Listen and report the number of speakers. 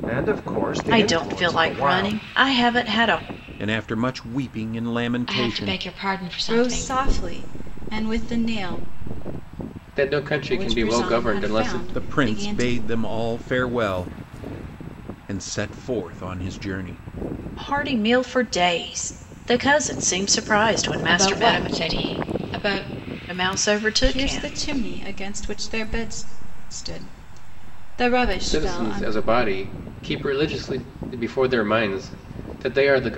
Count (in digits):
6